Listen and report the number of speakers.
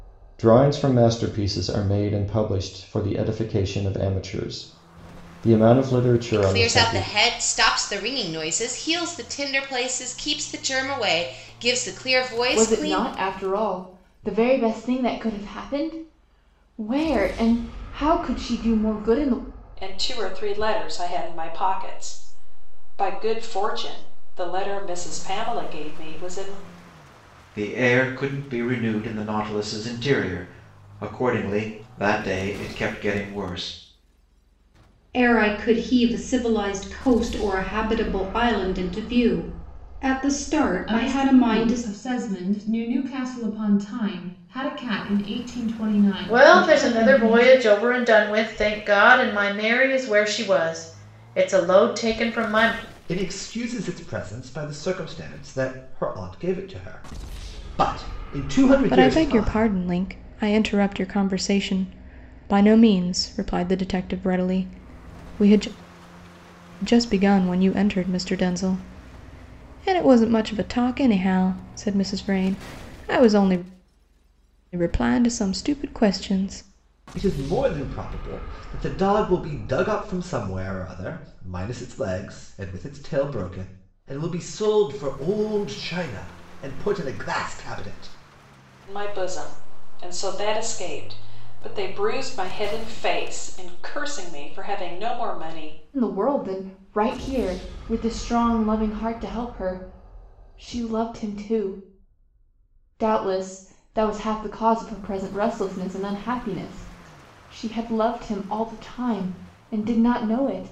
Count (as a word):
ten